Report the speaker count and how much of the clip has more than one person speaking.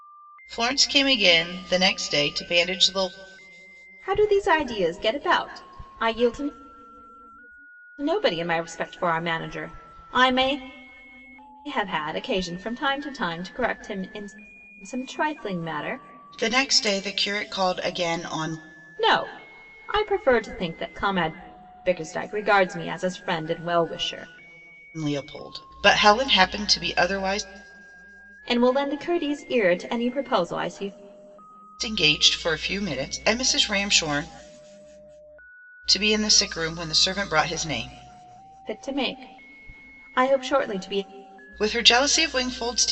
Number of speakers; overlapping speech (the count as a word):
two, no overlap